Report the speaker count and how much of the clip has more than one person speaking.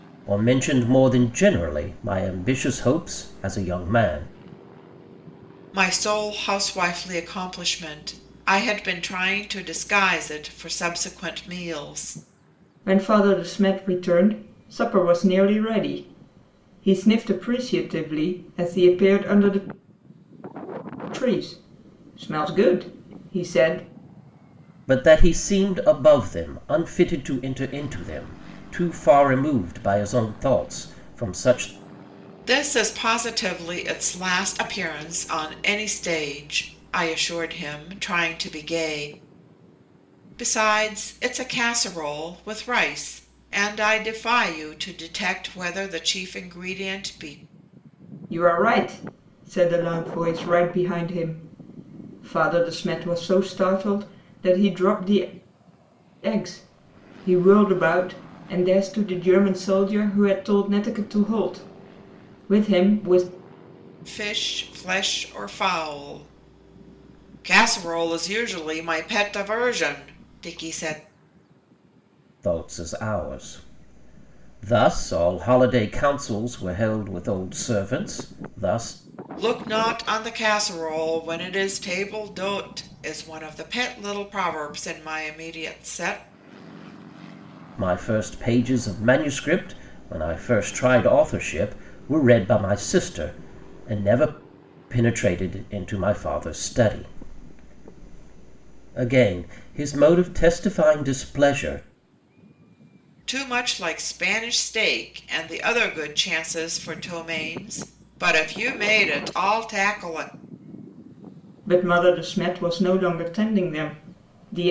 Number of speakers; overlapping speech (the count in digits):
3, no overlap